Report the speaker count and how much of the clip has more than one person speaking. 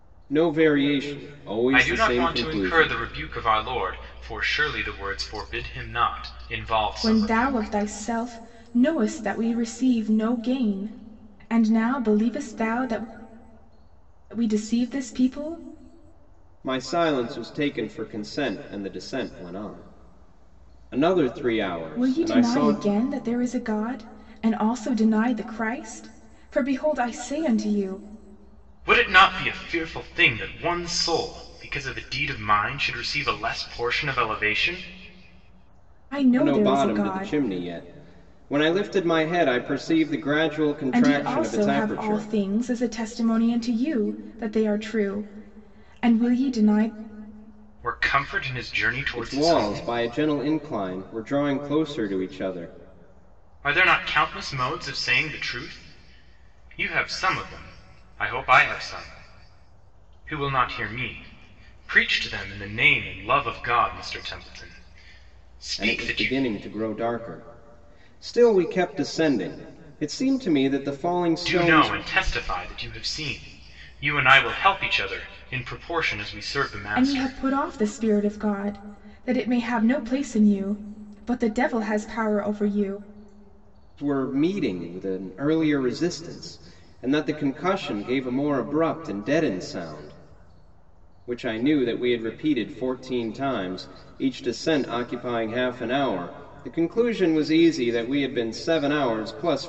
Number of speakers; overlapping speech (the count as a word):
three, about 8%